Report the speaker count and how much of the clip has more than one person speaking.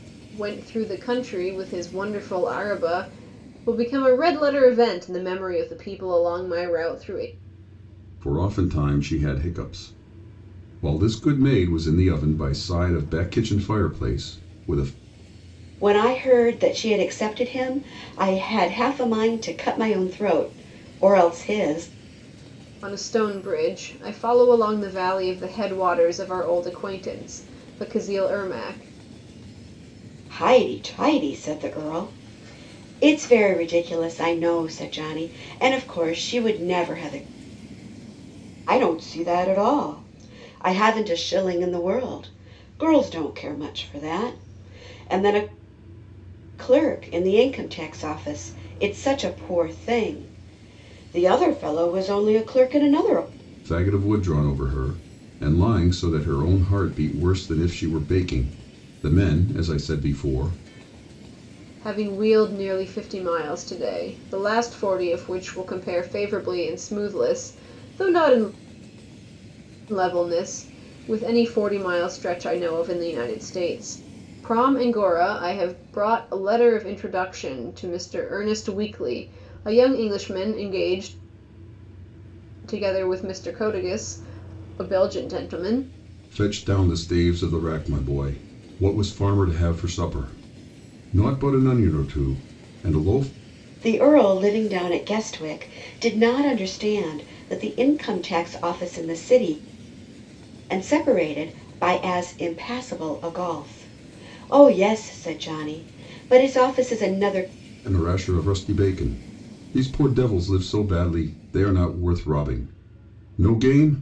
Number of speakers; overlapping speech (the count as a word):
three, no overlap